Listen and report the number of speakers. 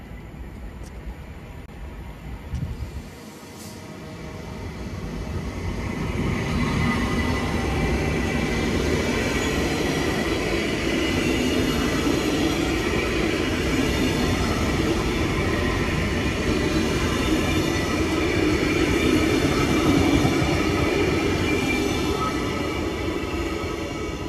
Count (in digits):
0